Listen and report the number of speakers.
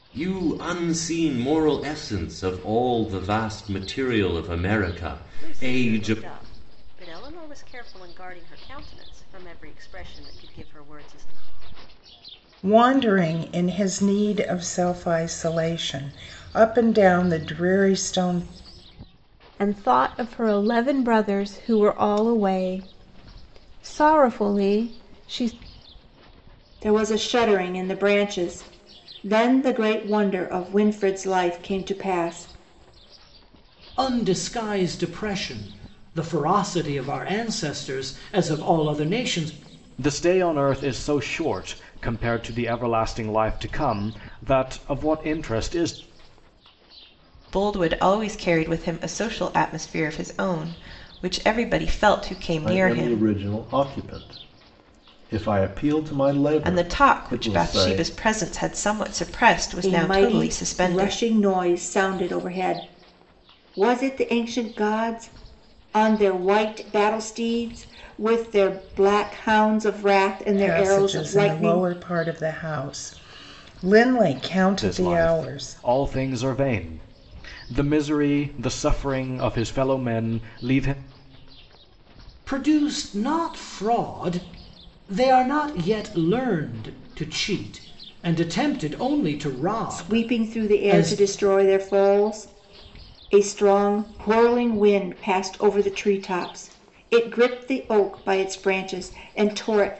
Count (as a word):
nine